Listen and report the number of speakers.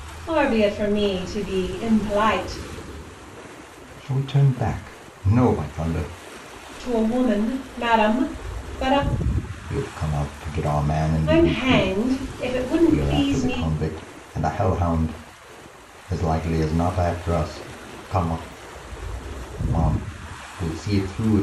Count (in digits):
2